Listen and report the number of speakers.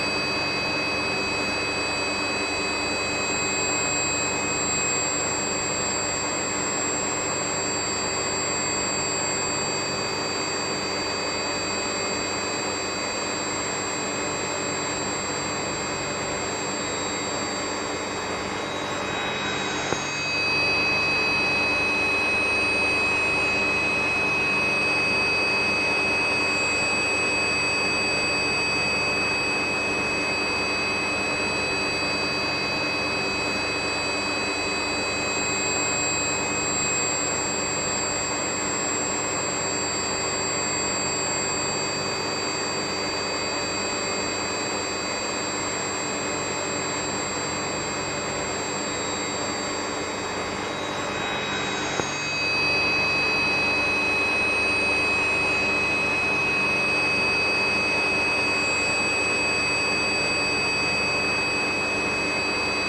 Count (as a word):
zero